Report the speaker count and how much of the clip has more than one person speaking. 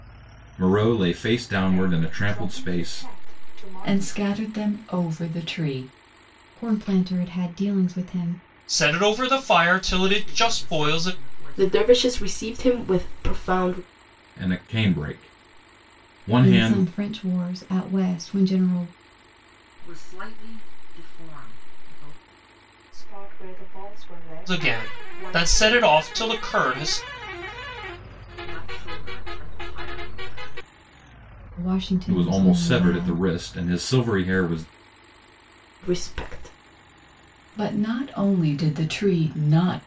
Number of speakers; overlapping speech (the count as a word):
seven, about 15%